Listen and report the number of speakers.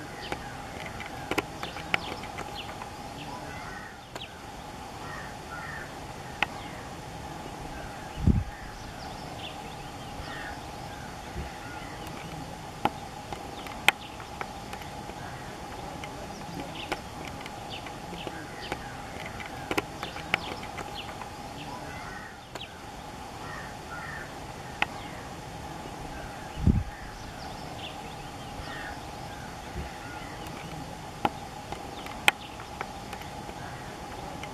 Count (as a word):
zero